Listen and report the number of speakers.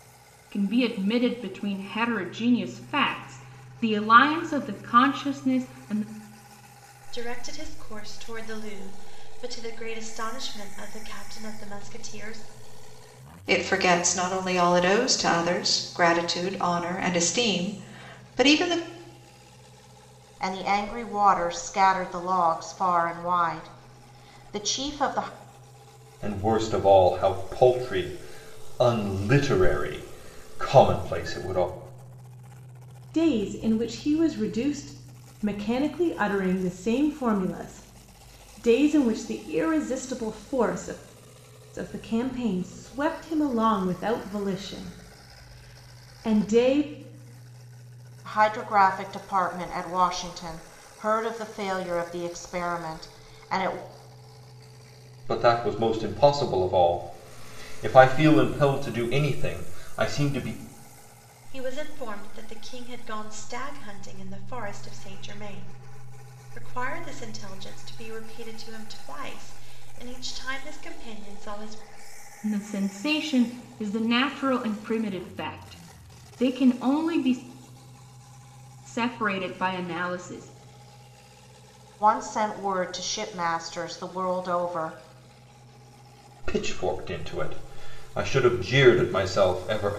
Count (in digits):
6